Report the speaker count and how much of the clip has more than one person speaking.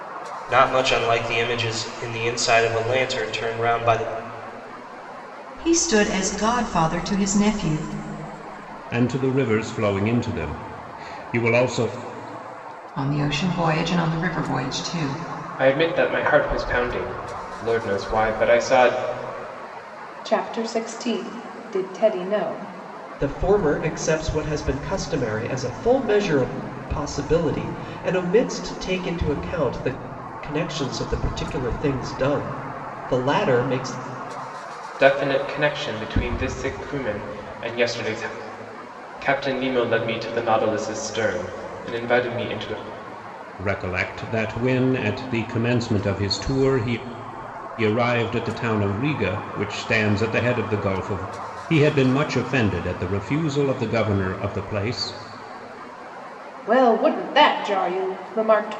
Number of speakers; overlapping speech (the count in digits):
7, no overlap